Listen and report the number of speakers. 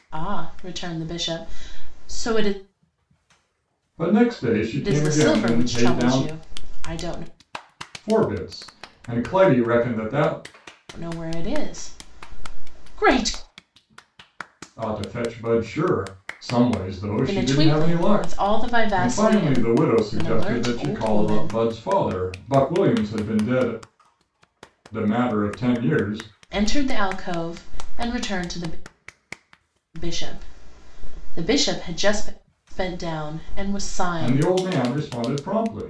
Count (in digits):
2